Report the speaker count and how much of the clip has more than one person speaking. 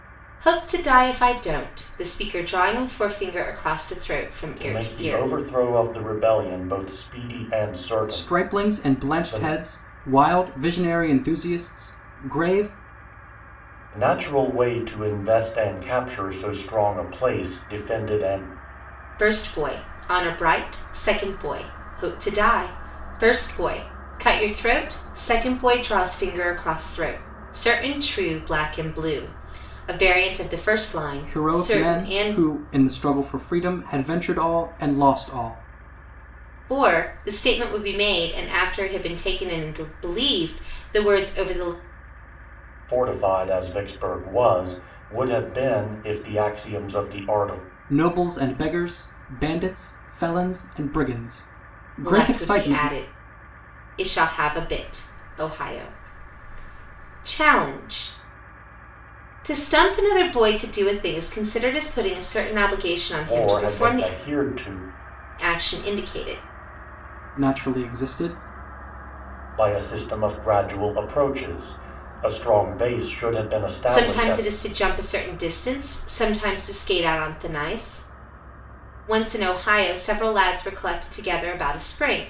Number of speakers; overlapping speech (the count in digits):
3, about 7%